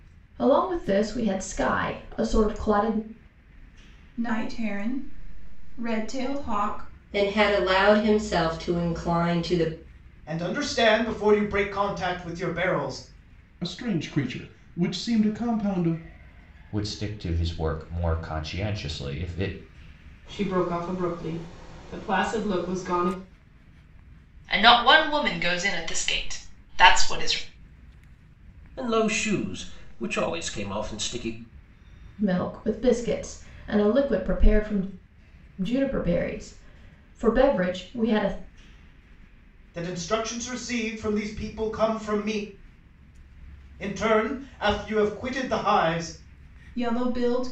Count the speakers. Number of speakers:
nine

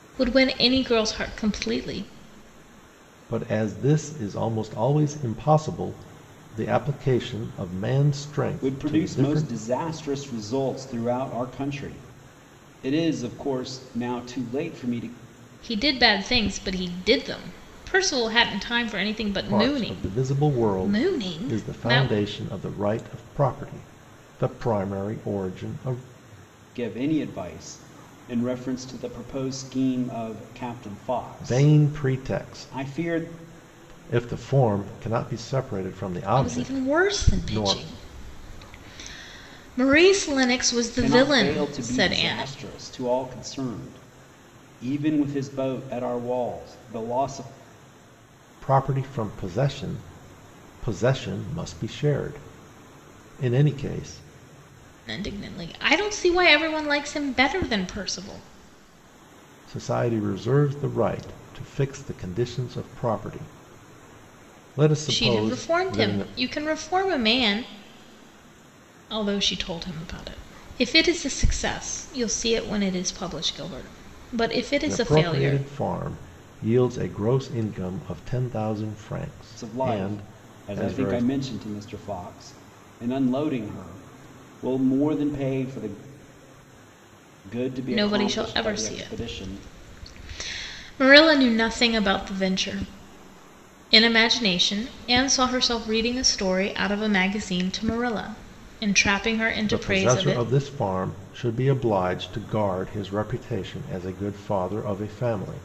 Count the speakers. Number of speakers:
three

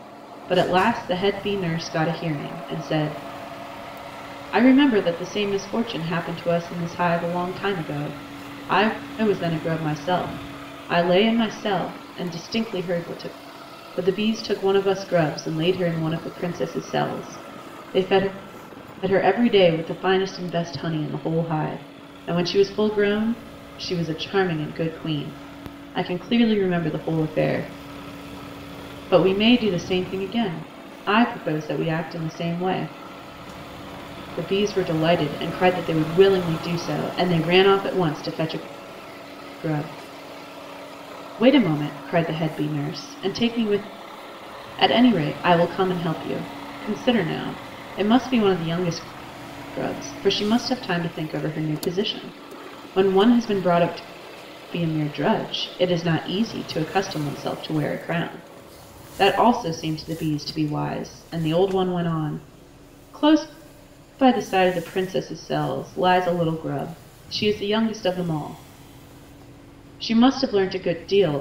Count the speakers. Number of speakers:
one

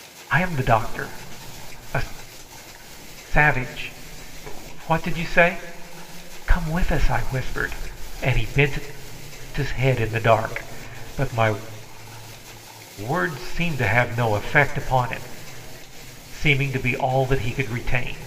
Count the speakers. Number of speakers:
one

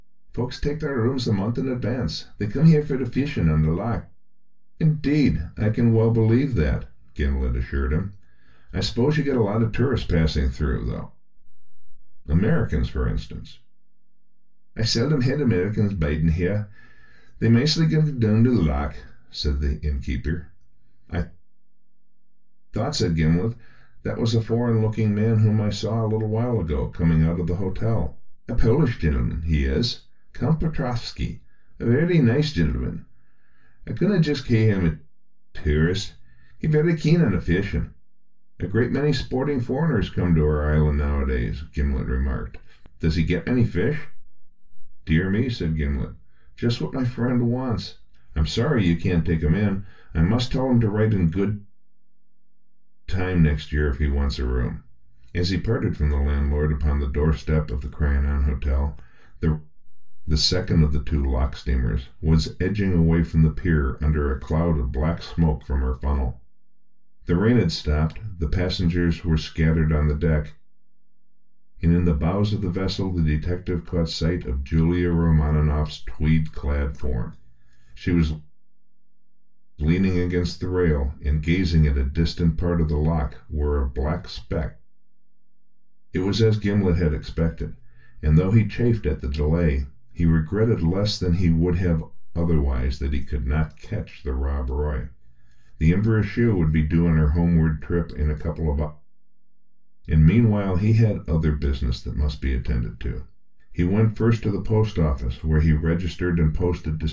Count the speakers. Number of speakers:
one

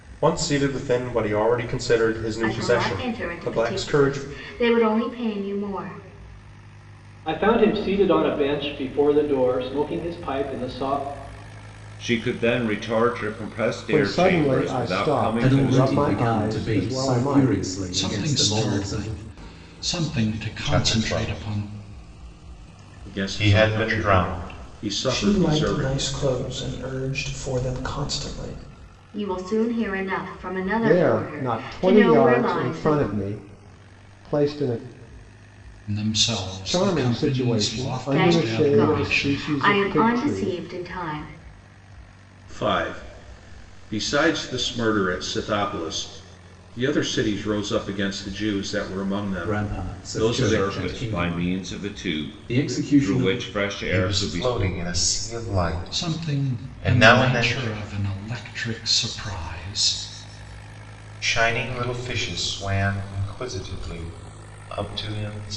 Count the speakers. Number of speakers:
ten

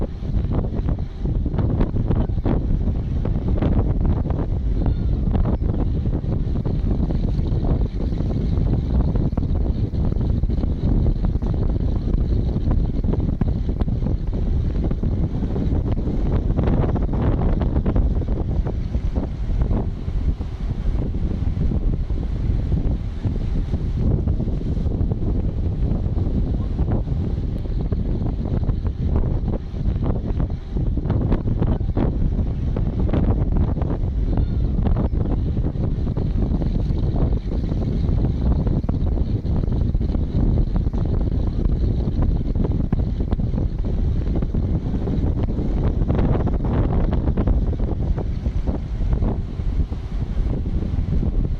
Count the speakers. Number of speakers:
zero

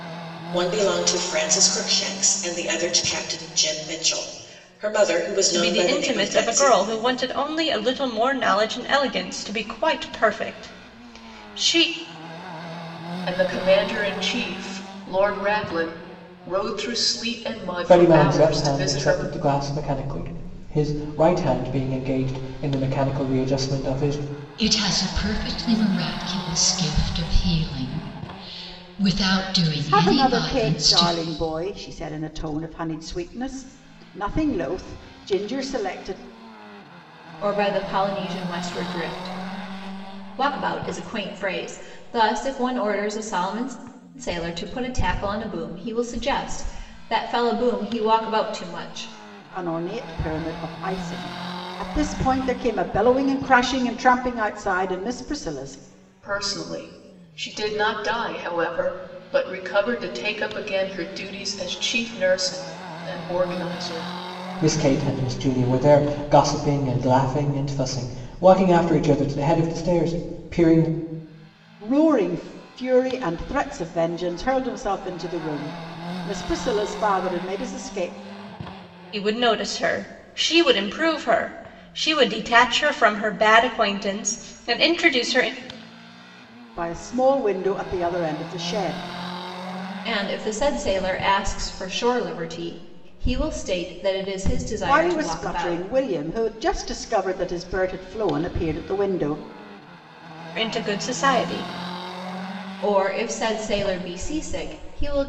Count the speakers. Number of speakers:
seven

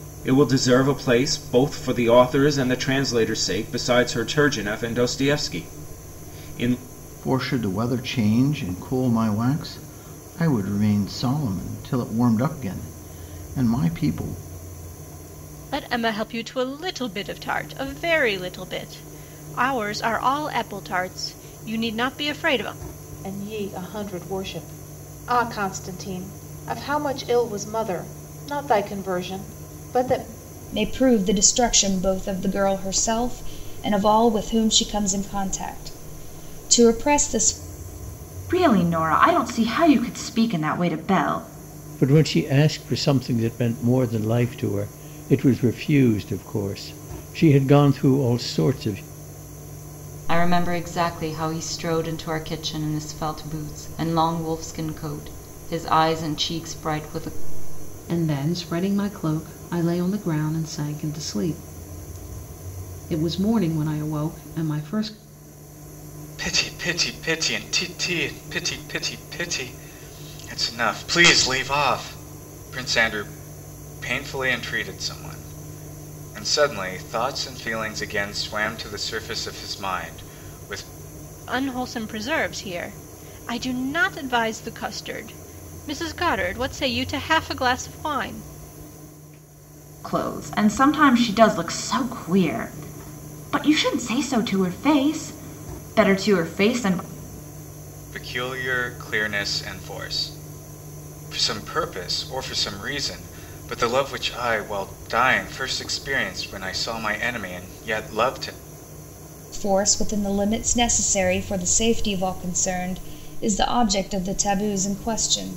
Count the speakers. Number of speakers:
ten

